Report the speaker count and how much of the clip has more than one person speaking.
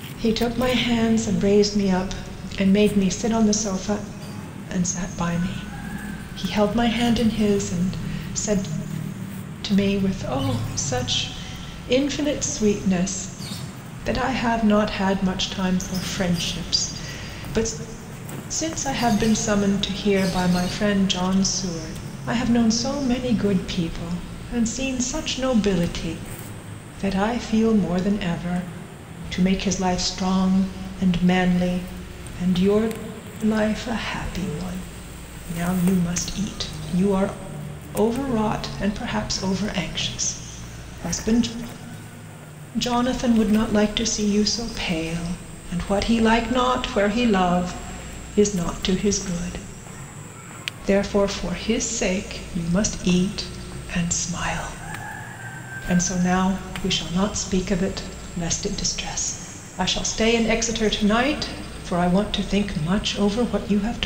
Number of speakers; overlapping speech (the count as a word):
one, no overlap